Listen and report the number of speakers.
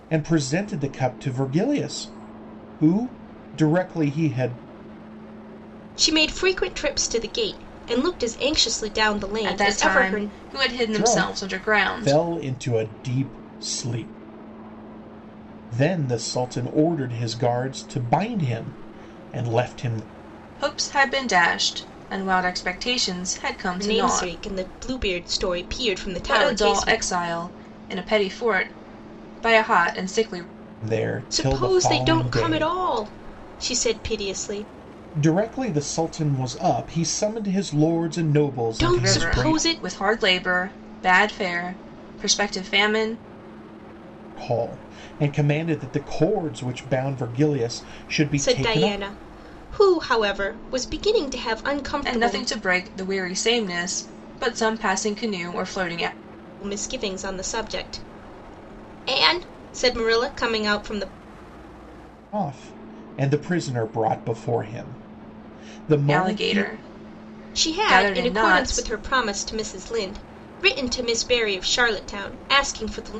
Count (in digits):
3